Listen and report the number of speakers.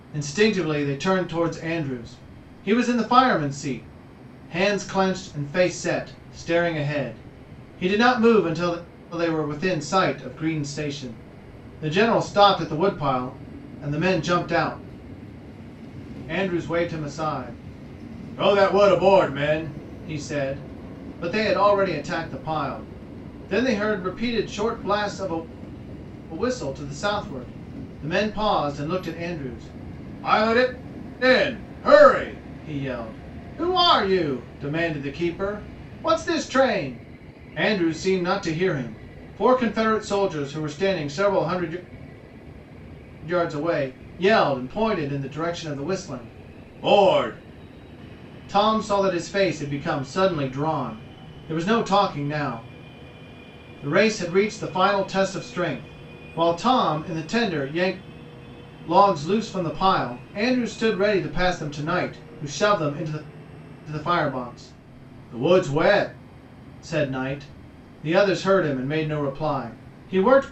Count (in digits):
1